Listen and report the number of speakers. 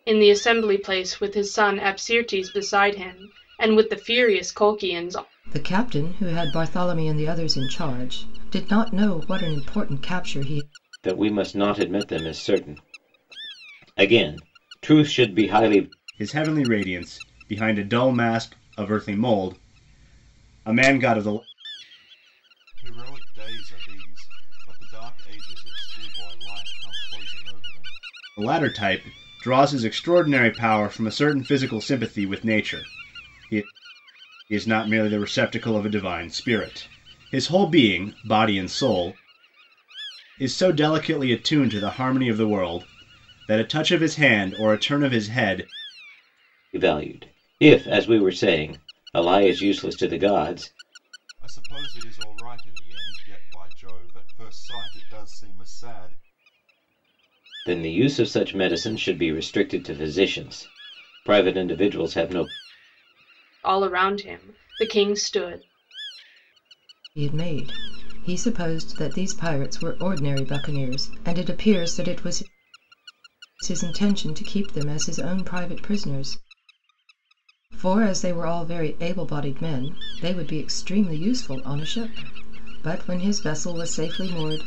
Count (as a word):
five